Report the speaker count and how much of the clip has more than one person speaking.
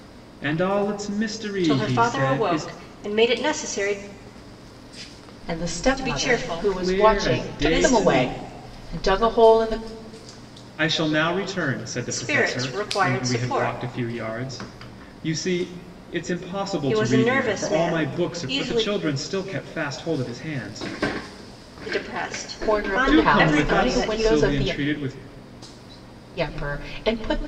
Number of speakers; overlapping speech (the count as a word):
three, about 35%